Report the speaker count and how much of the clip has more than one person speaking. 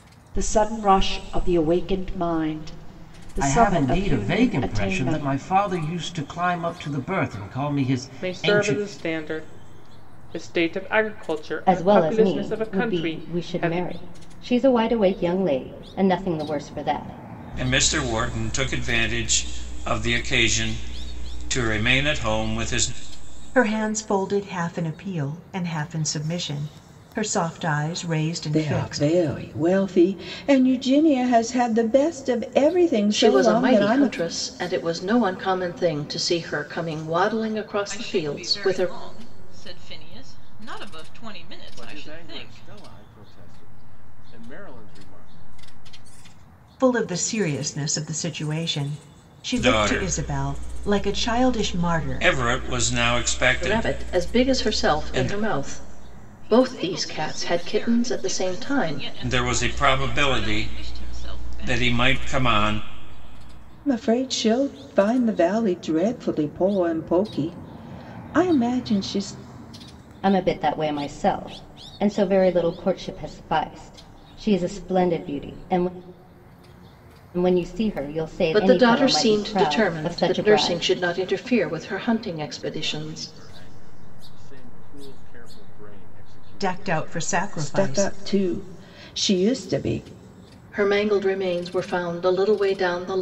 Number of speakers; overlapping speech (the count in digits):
10, about 25%